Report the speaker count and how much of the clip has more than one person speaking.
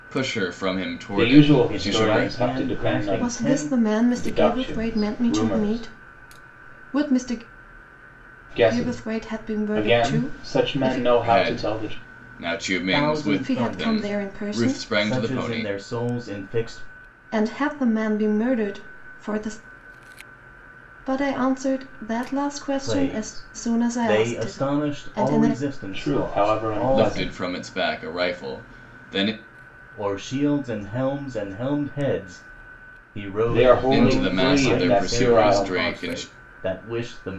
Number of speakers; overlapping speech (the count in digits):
4, about 44%